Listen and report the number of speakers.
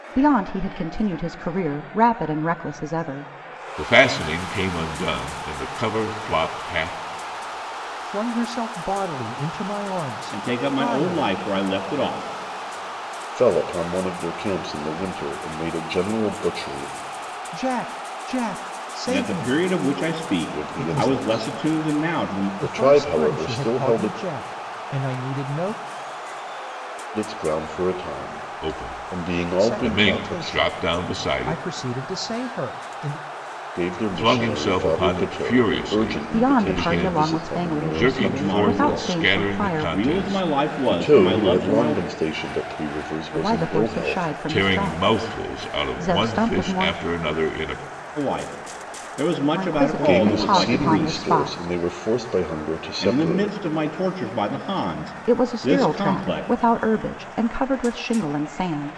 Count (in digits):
5